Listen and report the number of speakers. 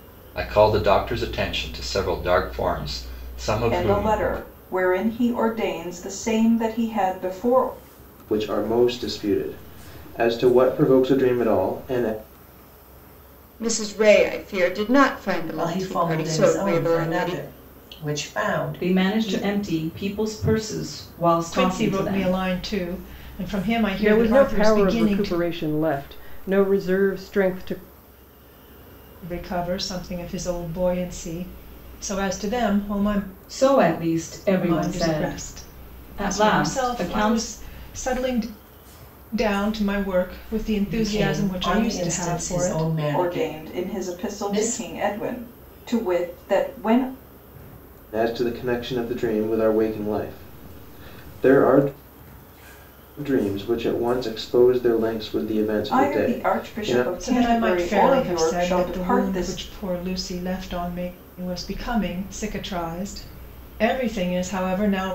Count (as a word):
eight